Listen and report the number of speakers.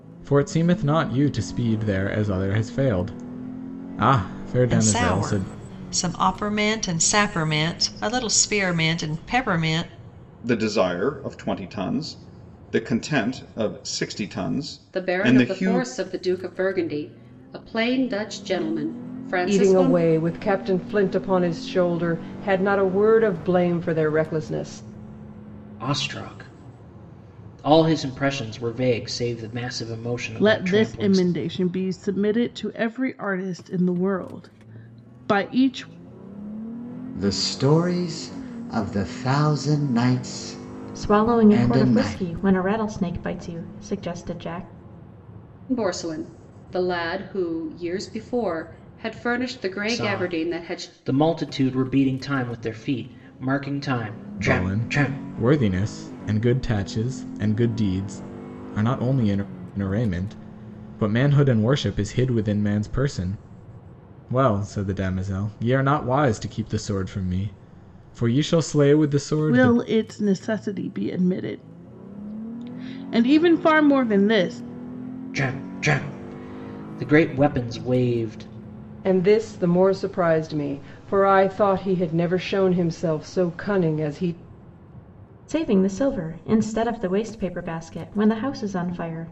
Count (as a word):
nine